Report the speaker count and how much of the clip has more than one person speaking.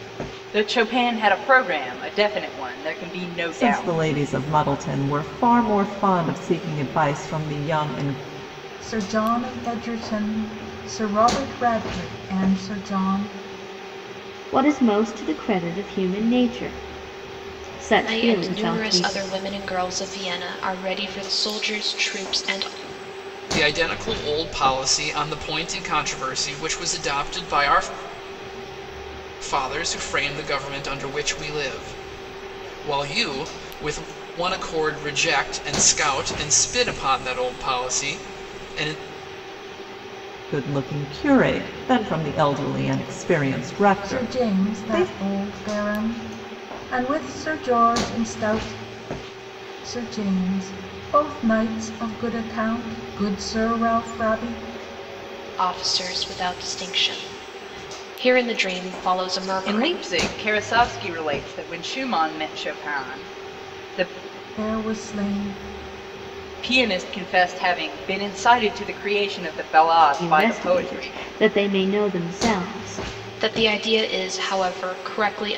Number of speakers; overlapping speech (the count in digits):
6, about 5%